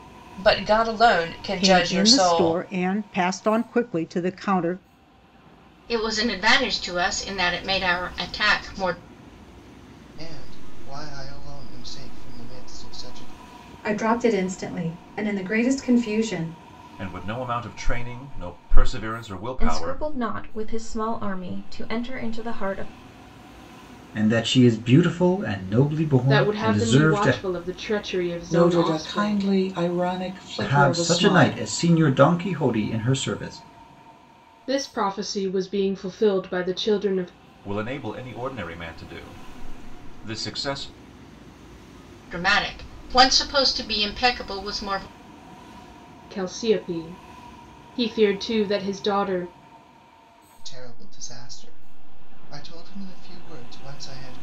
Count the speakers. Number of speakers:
ten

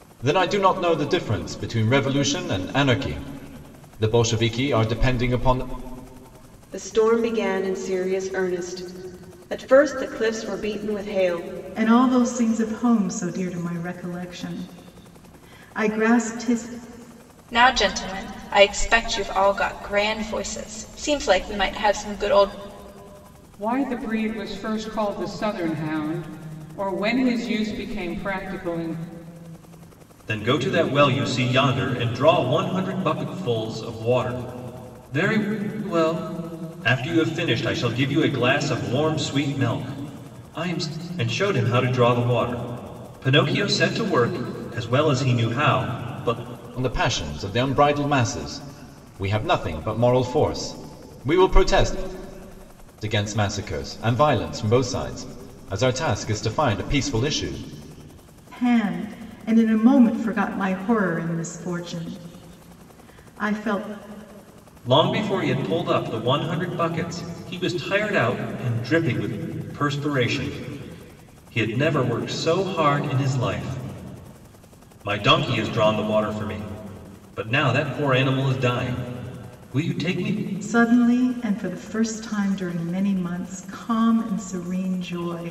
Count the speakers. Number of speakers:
six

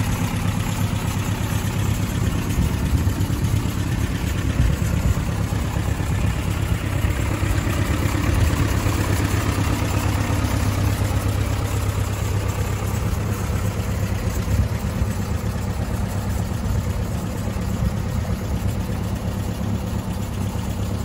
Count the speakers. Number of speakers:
zero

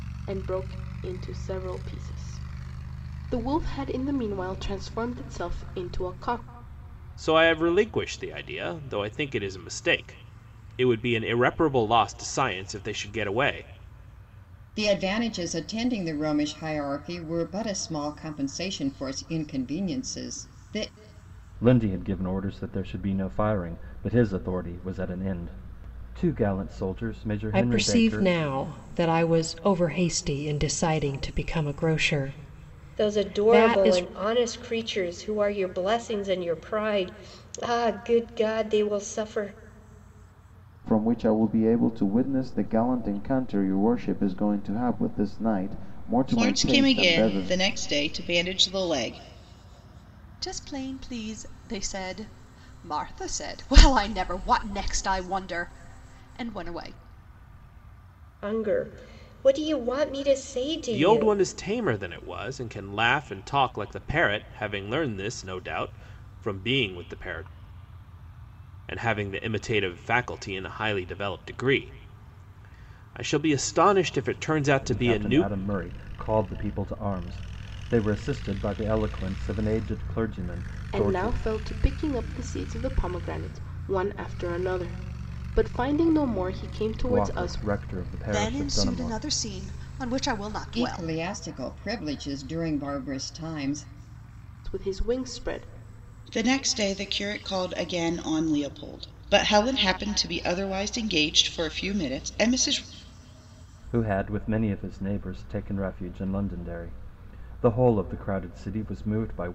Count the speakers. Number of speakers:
nine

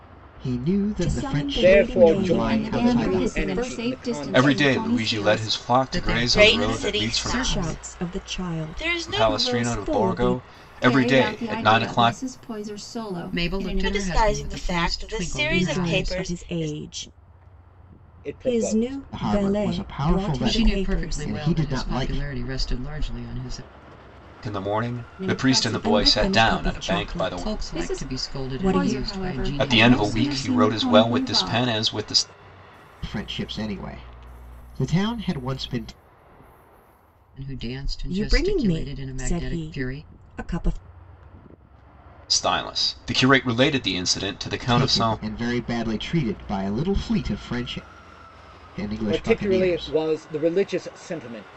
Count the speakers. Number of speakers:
seven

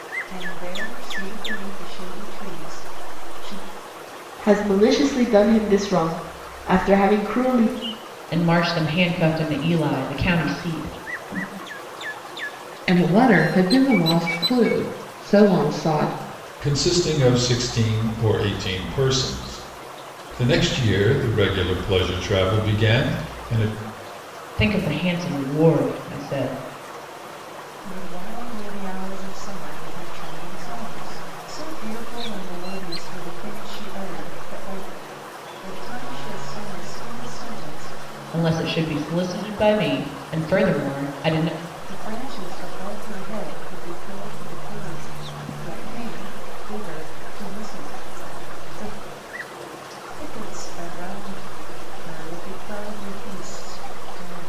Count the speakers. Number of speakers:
five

